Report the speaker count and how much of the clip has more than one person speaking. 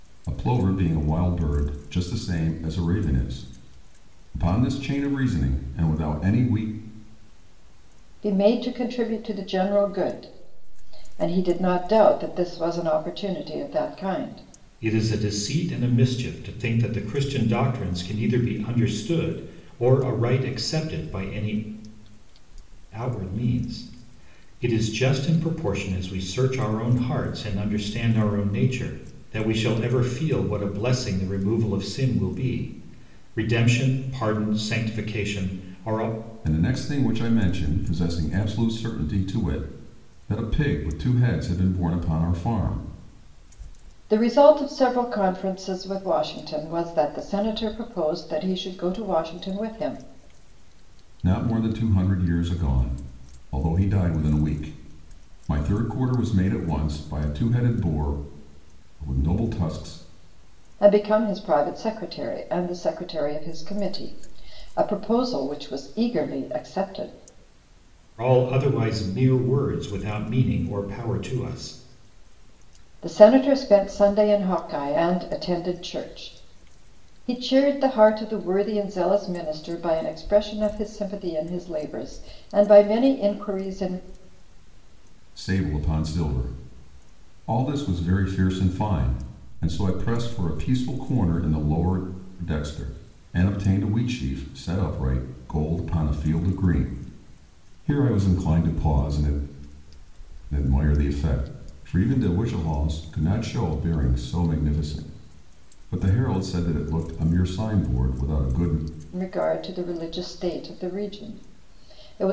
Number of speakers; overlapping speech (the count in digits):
3, no overlap